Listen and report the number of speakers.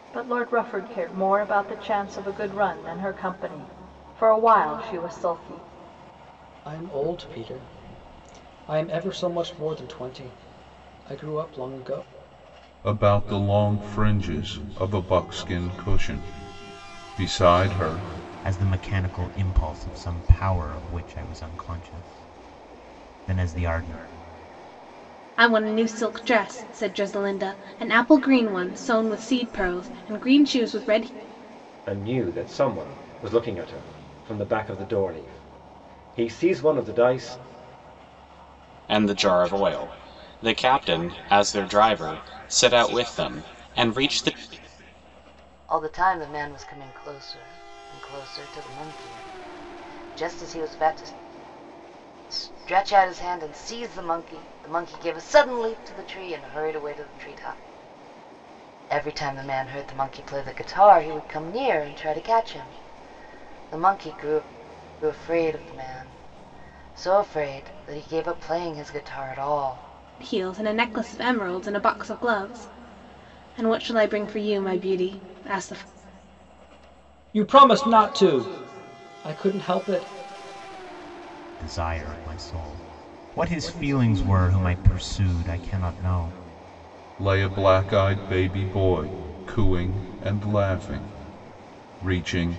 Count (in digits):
8